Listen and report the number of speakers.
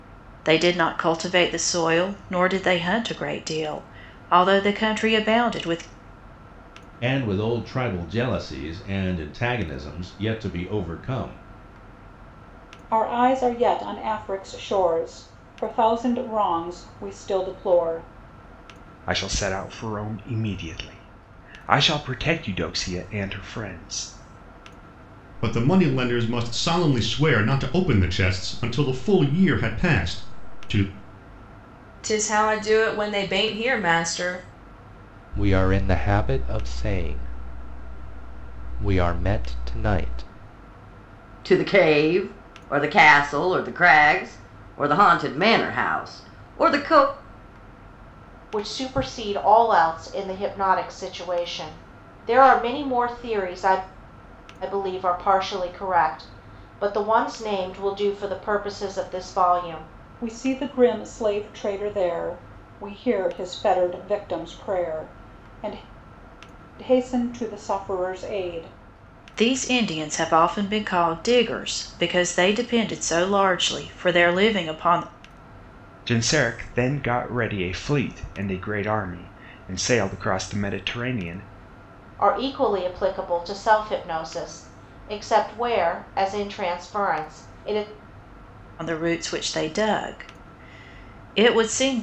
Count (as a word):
nine